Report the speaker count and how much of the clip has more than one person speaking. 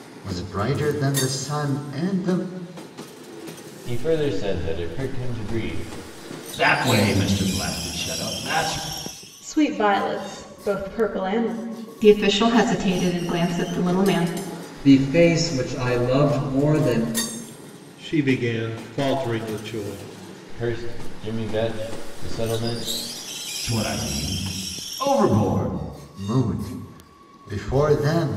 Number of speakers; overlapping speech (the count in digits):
7, no overlap